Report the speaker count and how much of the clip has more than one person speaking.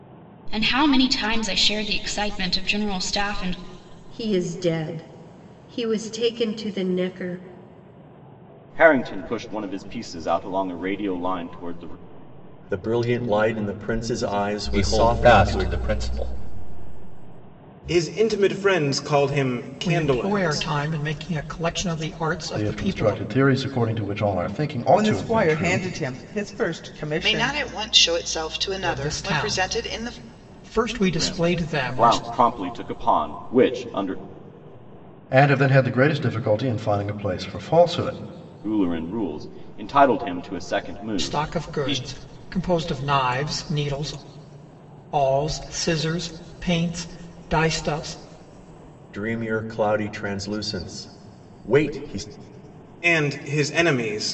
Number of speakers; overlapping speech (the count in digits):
10, about 14%